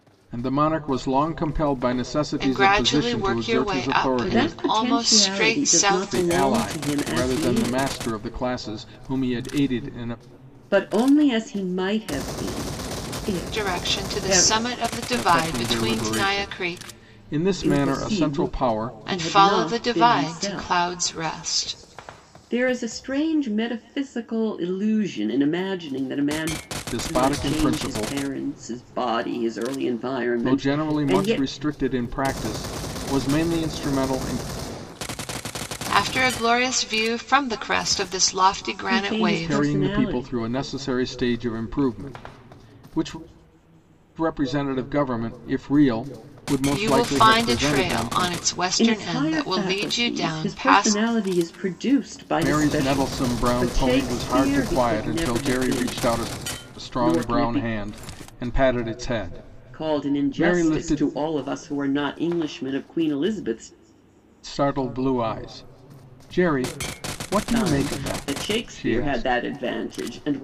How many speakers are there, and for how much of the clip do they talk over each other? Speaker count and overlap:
3, about 39%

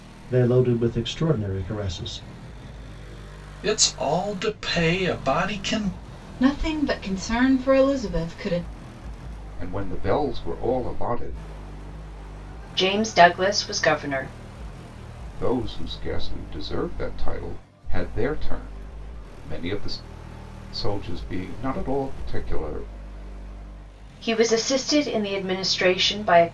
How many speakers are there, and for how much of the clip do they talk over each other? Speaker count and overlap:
5, no overlap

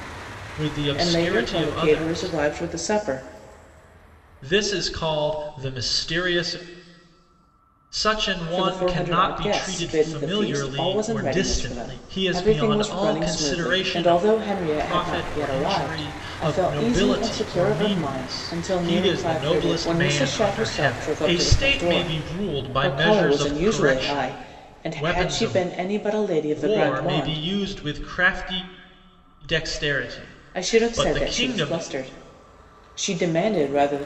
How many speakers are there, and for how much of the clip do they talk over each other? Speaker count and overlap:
2, about 58%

